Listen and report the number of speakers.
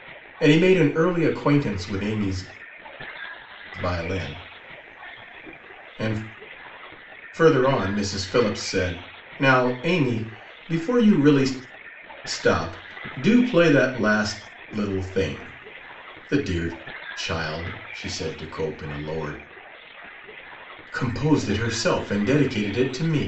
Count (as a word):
one